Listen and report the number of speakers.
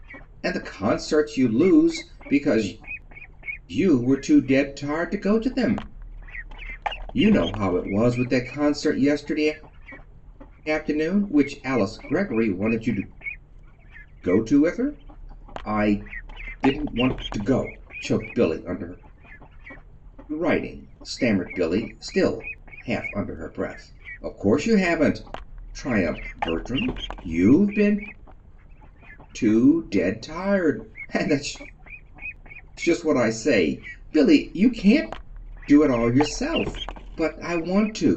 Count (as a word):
one